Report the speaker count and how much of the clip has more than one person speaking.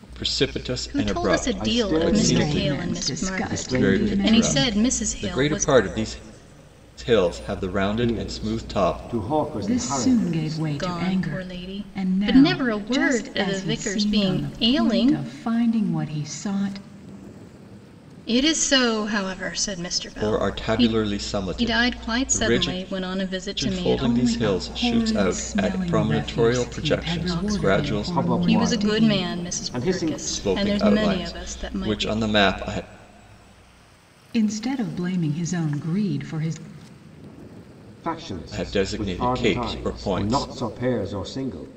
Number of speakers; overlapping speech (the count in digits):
4, about 56%